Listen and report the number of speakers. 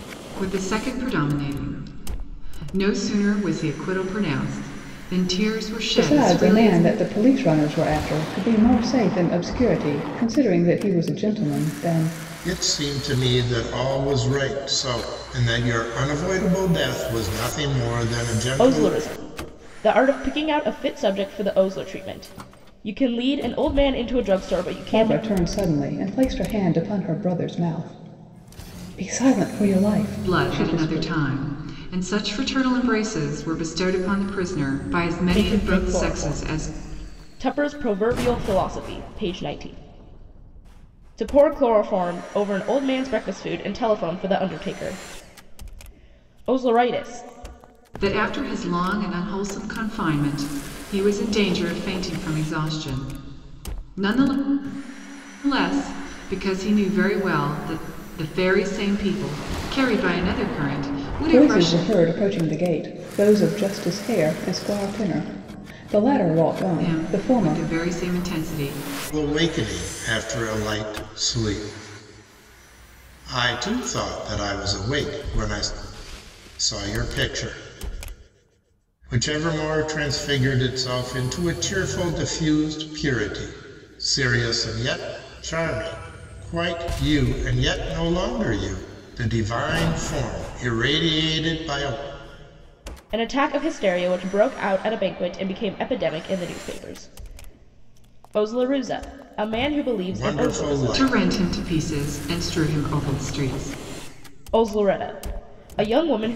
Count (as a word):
four